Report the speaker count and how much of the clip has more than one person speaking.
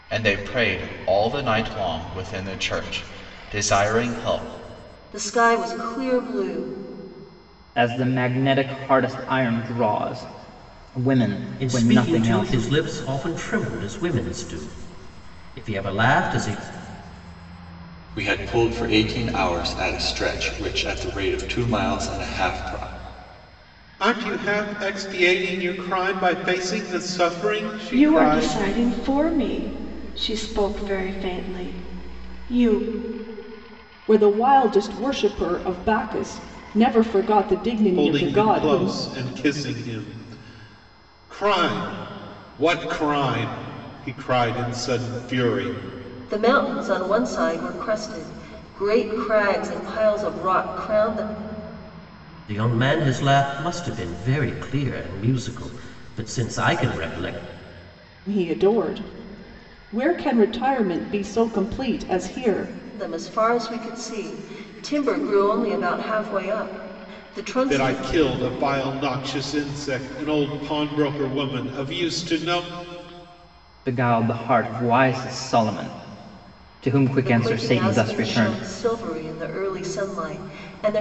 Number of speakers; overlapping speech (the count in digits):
8, about 6%